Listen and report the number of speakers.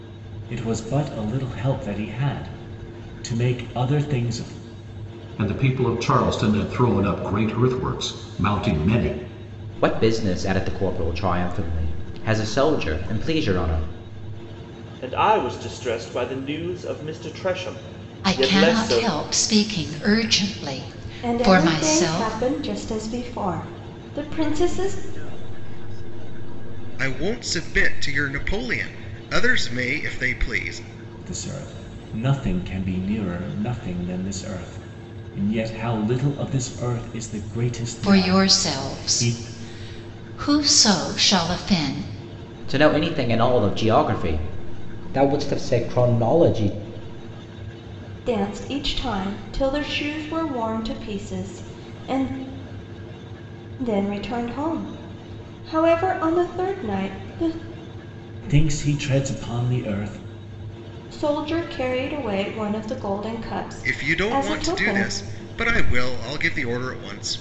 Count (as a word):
eight